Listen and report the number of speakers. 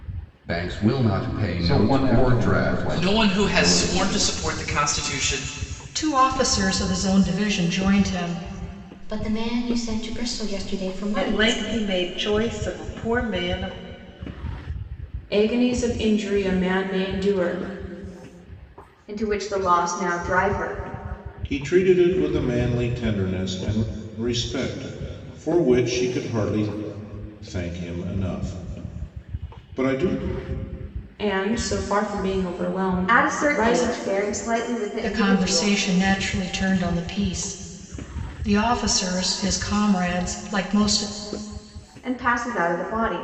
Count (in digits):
9